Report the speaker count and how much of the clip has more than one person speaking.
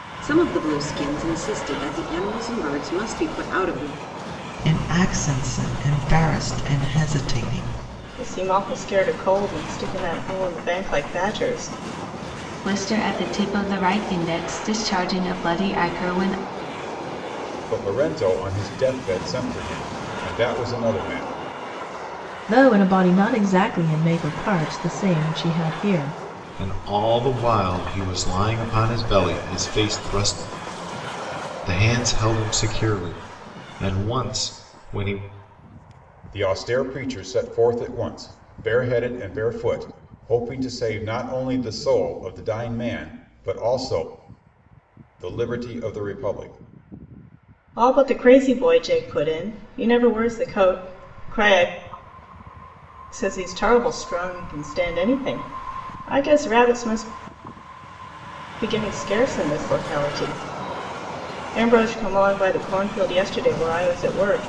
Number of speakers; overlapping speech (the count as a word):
seven, no overlap